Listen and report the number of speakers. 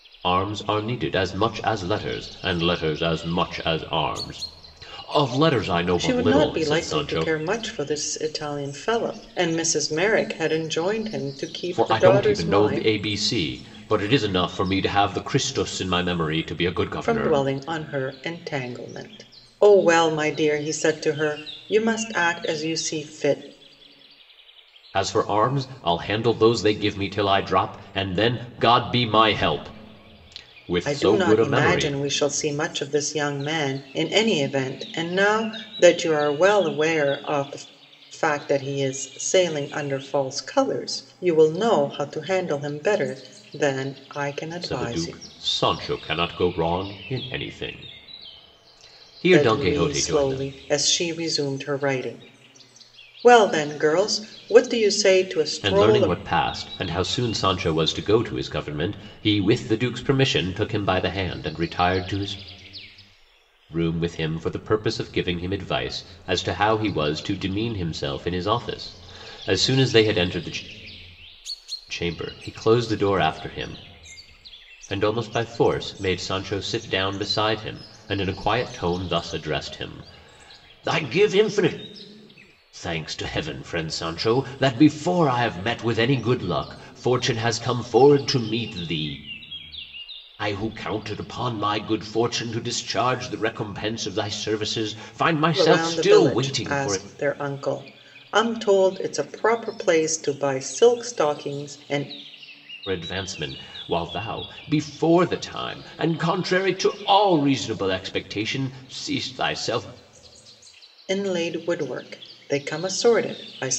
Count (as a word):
two